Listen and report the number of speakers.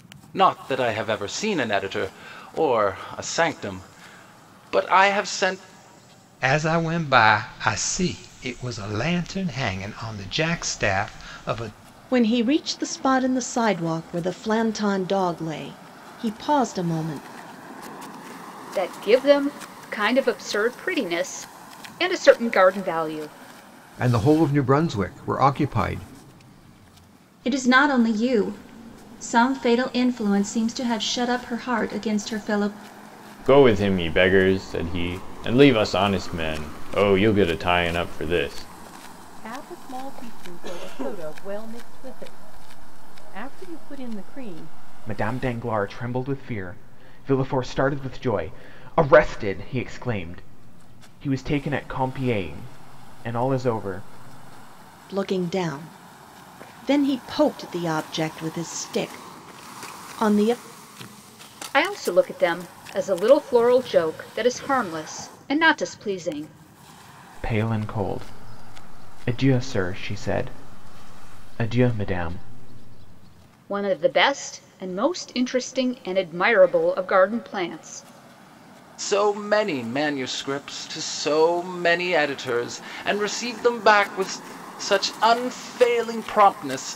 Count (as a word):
nine